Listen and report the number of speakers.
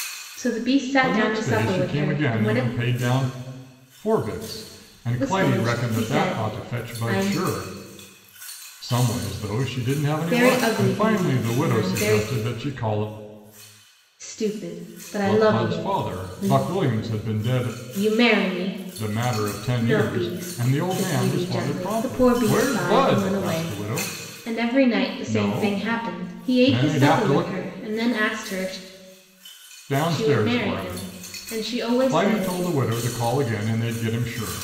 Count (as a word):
two